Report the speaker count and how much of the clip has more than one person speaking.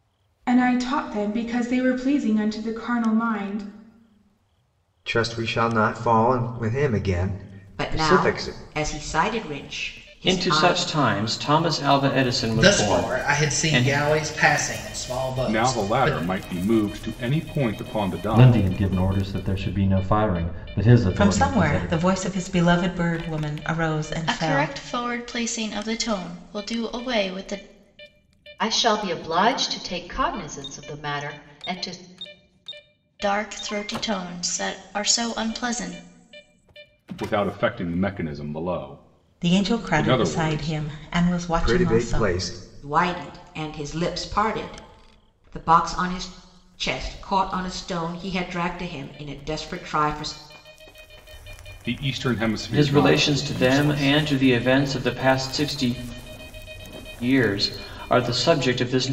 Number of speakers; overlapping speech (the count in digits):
10, about 15%